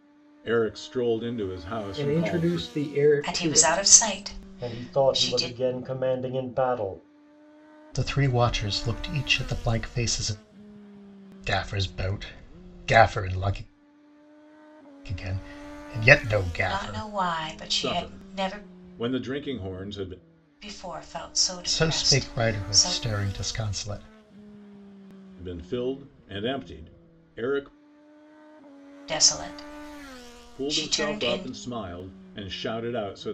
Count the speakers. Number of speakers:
5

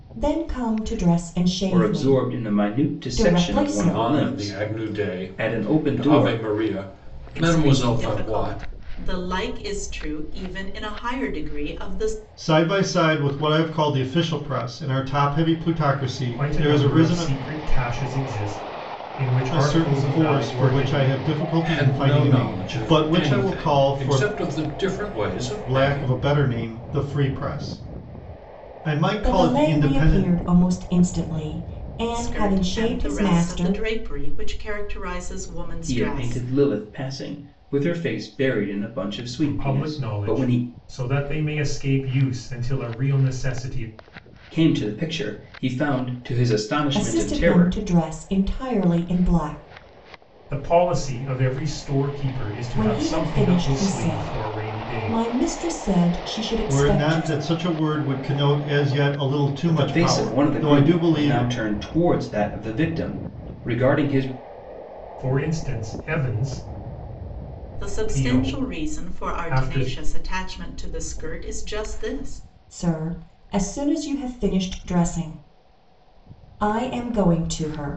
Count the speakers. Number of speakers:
6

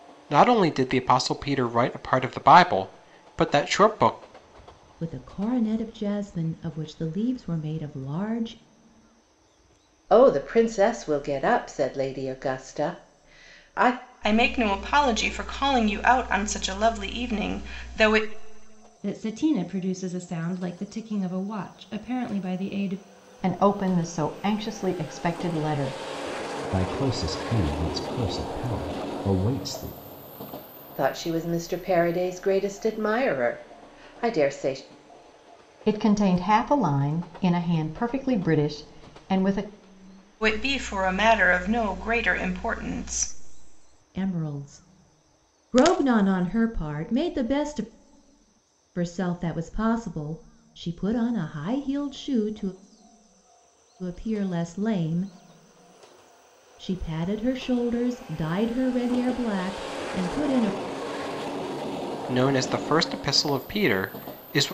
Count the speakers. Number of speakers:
7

